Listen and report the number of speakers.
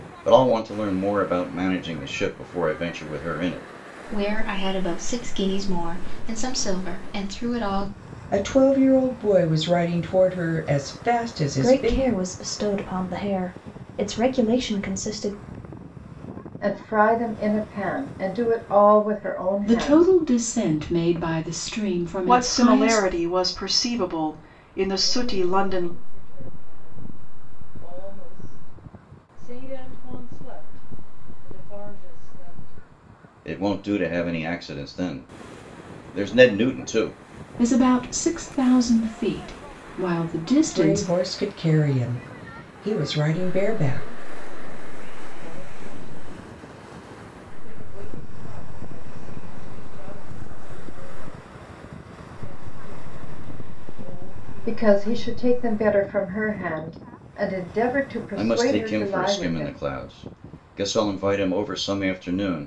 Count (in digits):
8